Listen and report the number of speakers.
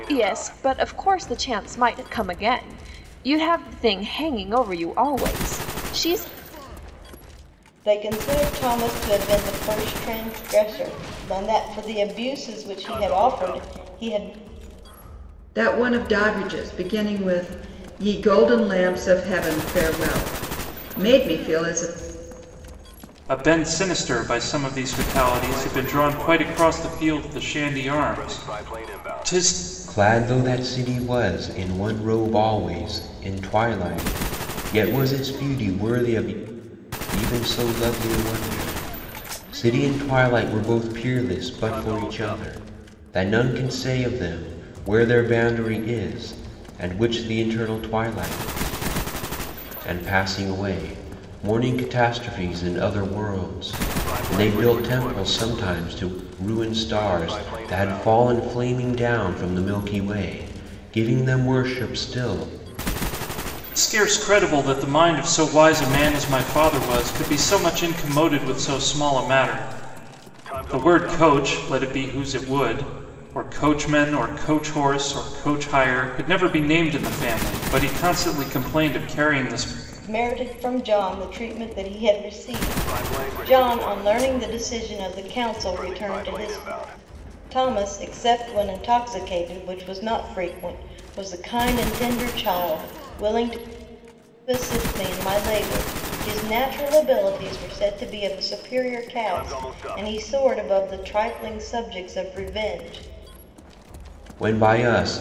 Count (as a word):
five